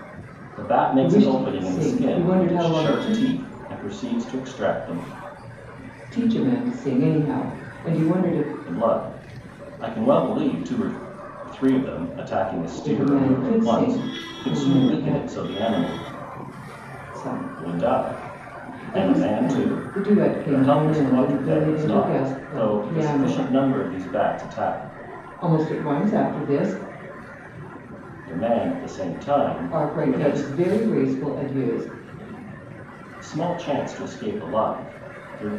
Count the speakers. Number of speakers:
two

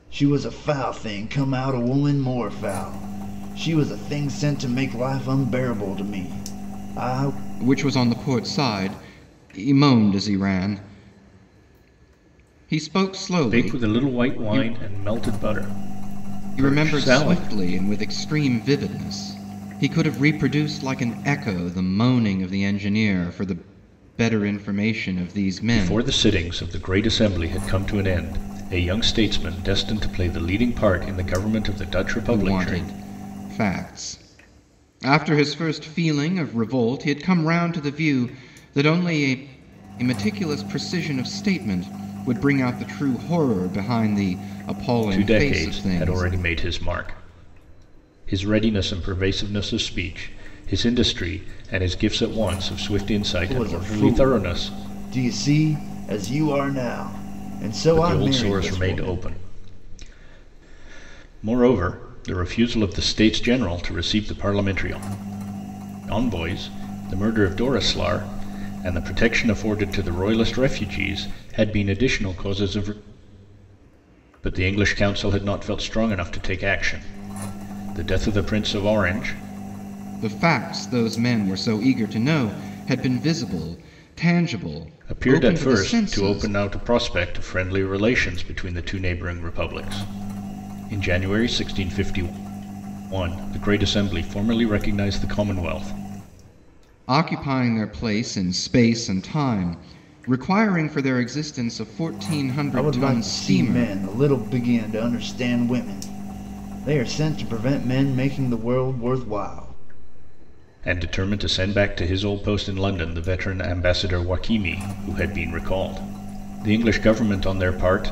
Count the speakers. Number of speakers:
three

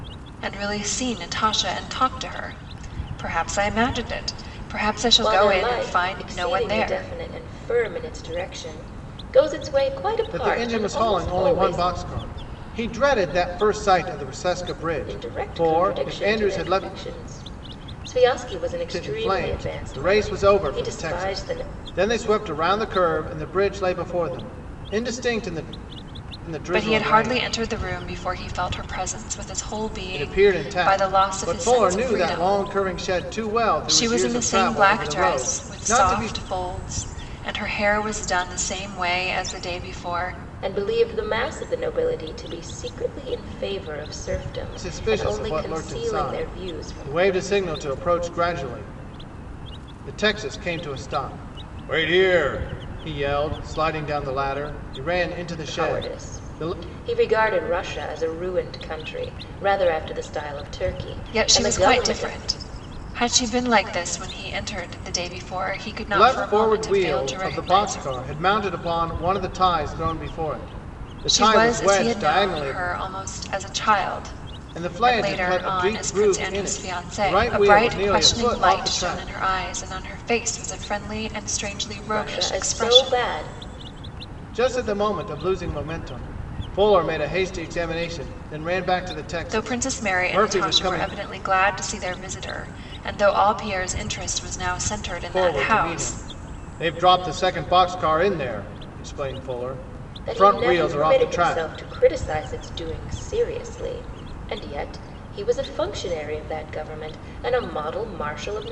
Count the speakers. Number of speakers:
three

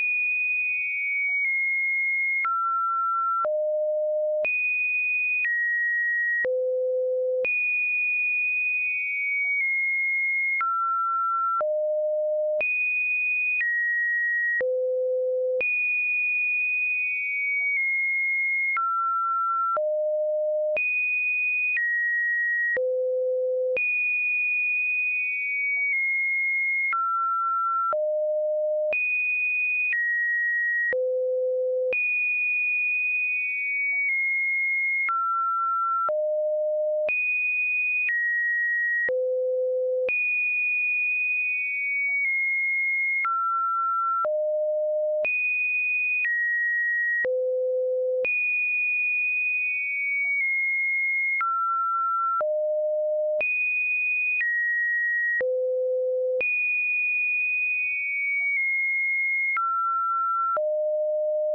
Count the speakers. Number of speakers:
zero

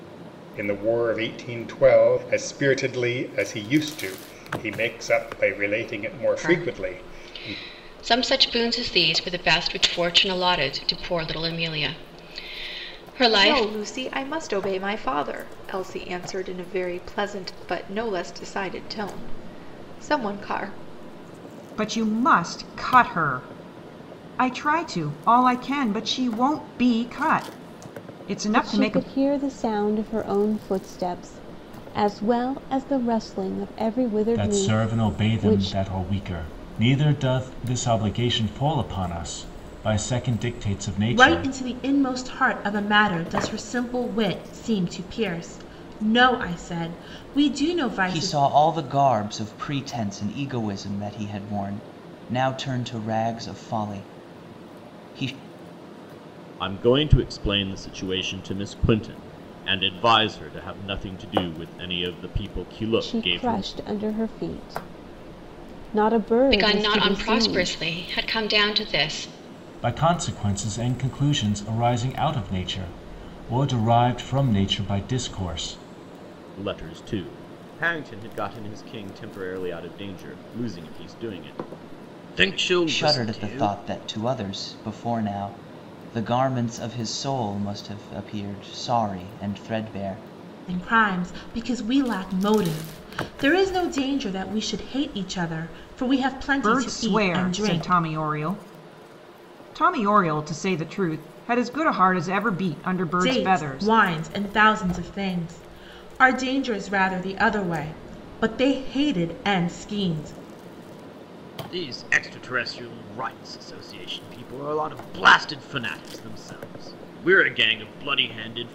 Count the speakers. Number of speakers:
nine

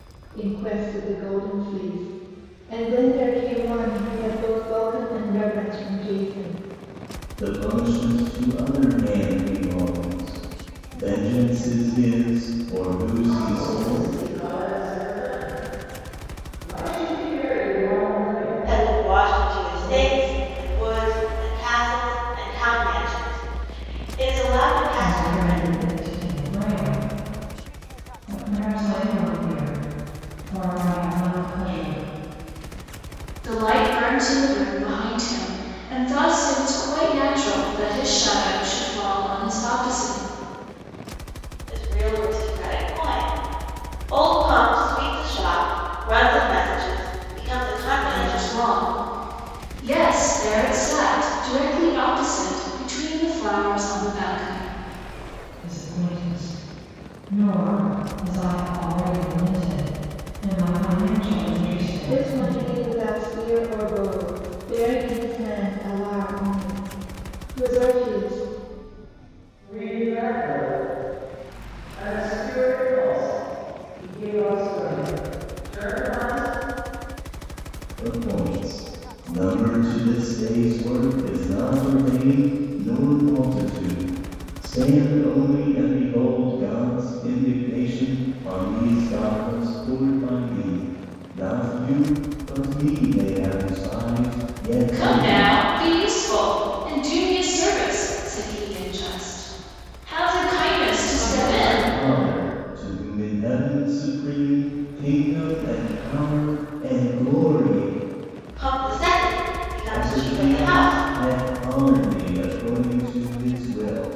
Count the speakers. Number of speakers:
six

